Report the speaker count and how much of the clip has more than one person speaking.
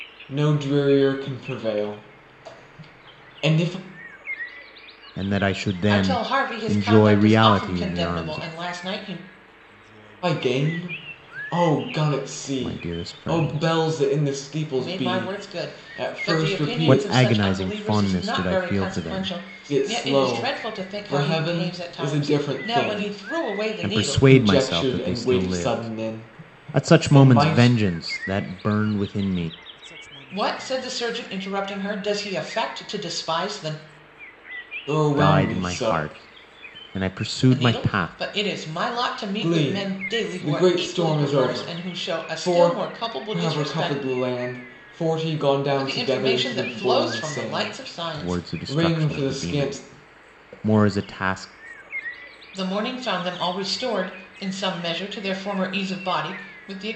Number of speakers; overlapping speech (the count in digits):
3, about 44%